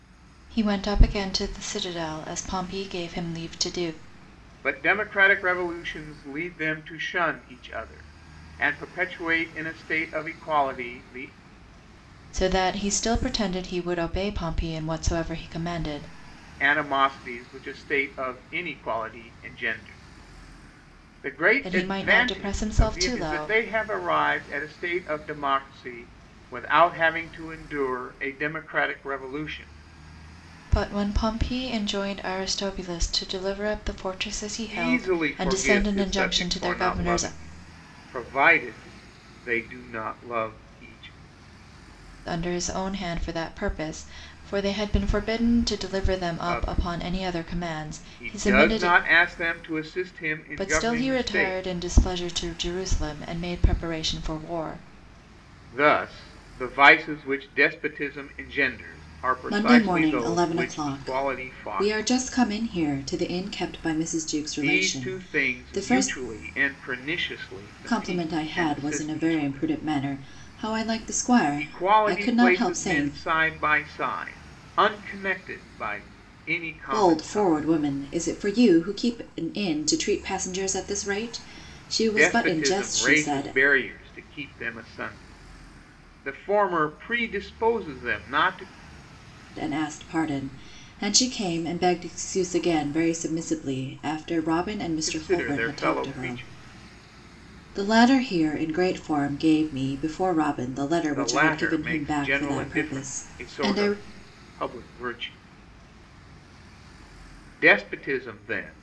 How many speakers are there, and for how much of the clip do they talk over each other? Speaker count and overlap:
2, about 21%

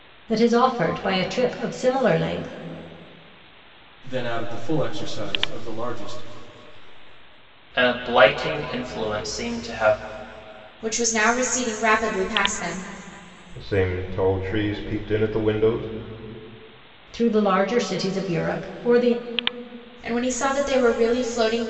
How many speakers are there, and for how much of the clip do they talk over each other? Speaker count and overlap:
5, no overlap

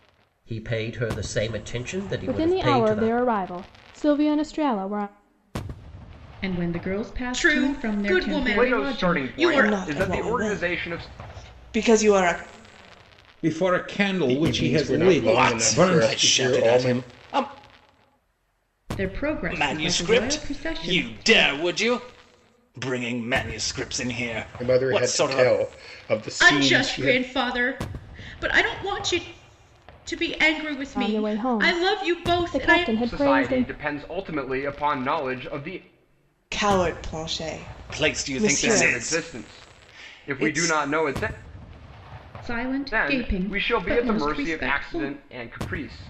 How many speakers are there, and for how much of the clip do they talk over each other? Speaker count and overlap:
9, about 42%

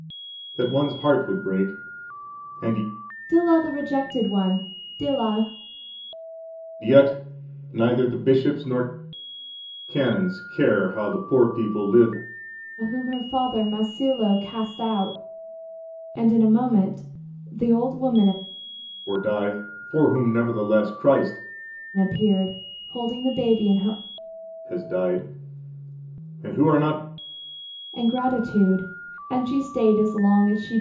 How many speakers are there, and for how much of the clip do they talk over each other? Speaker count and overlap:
2, no overlap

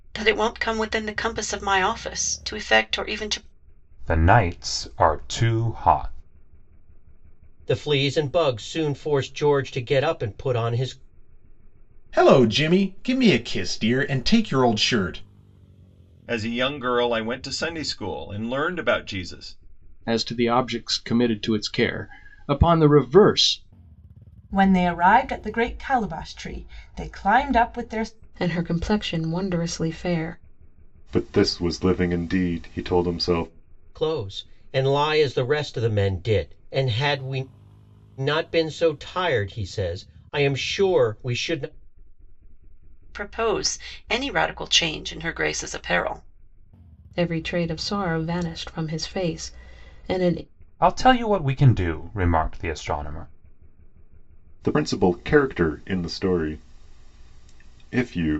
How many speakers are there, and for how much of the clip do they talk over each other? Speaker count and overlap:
9, no overlap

